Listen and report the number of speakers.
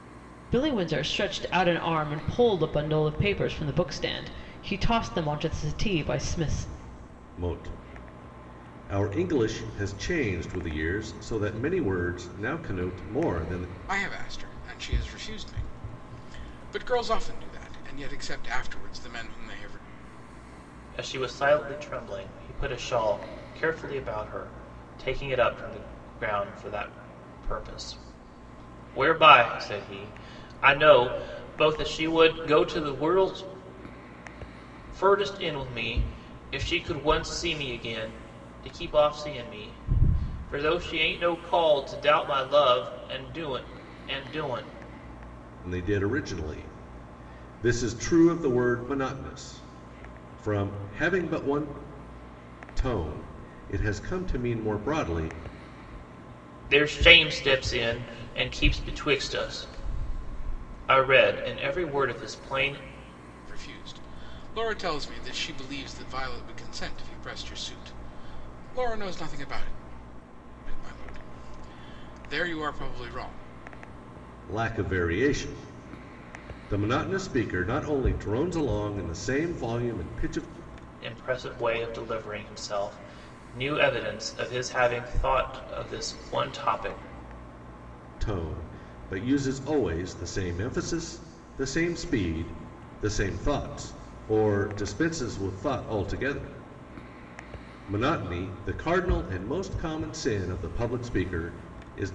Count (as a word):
four